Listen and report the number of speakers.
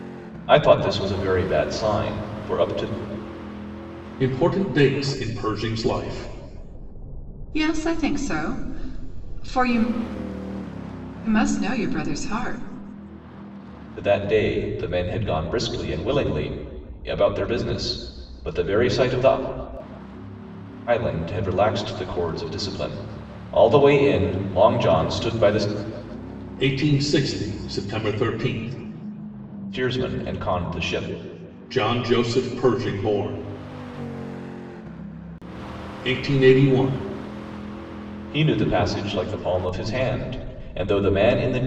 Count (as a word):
three